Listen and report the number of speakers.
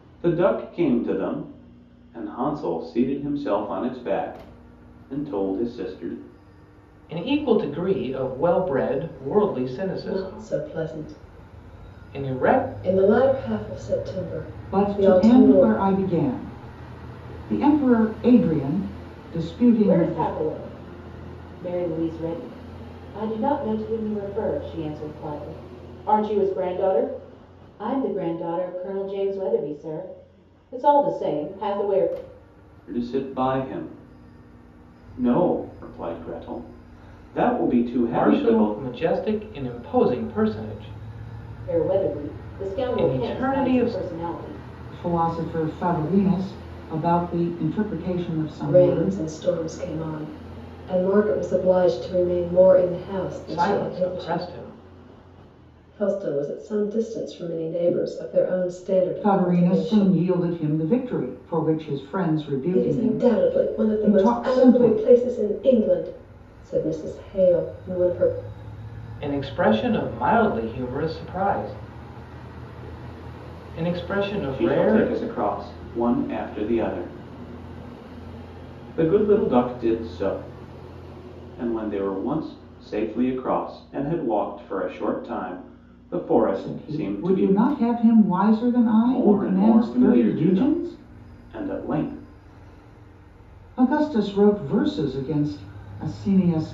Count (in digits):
5